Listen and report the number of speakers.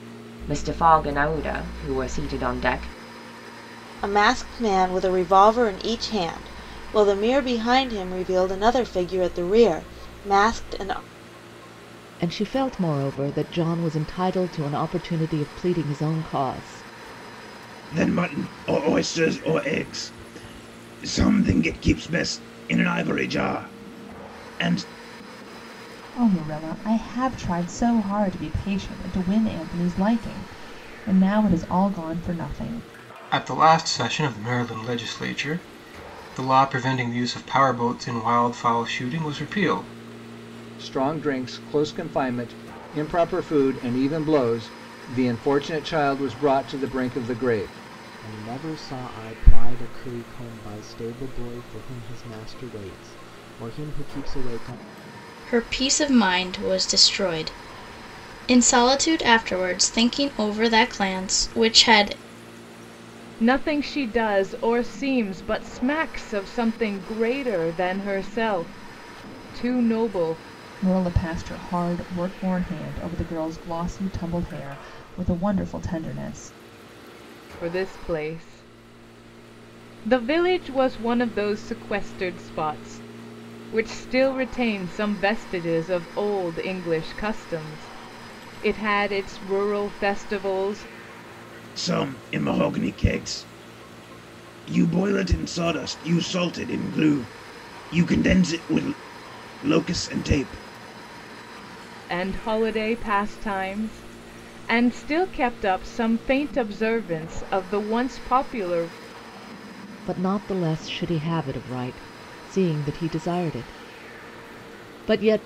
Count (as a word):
ten